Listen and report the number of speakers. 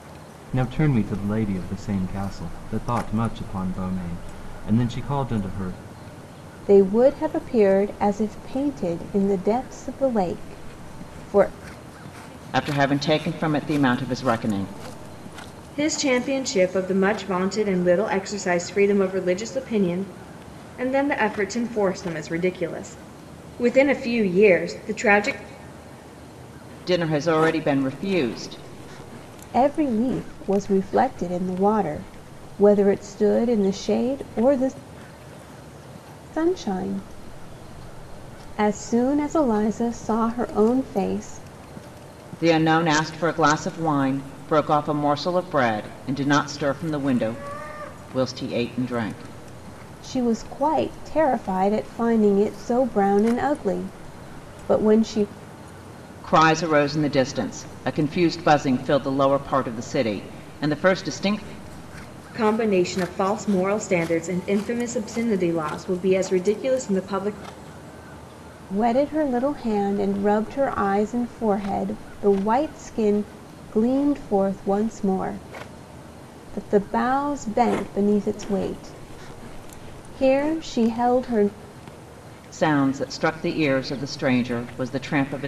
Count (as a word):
four